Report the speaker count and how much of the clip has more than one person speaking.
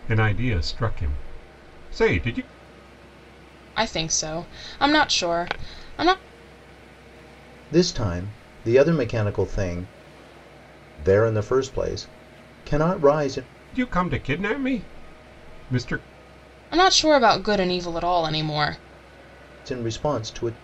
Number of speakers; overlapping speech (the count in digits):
3, no overlap